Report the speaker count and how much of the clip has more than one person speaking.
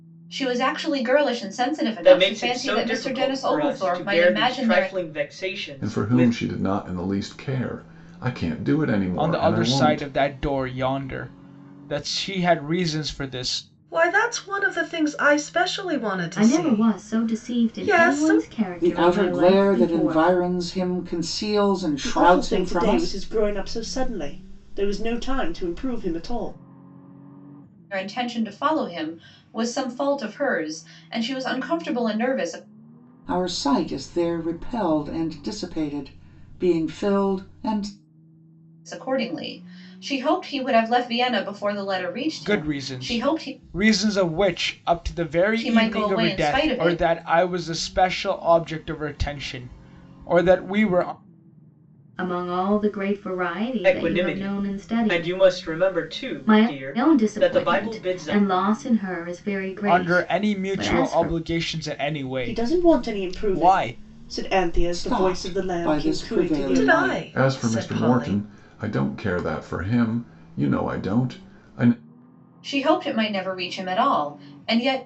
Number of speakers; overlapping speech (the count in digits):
8, about 30%